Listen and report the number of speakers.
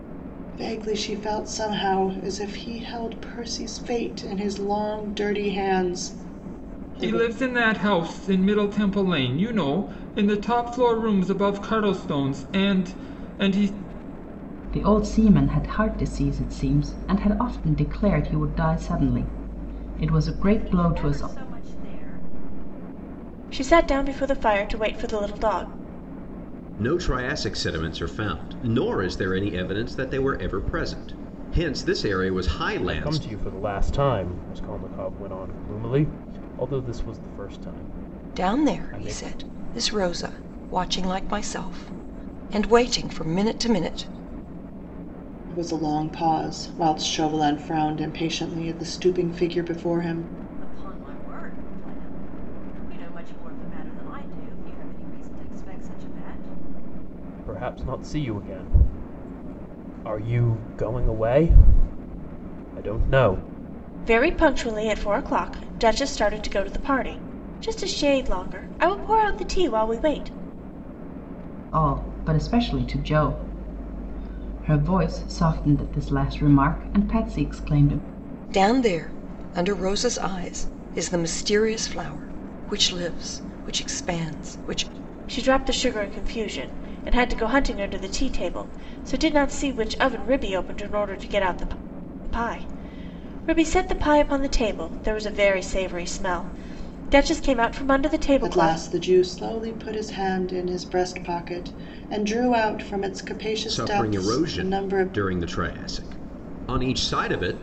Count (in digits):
8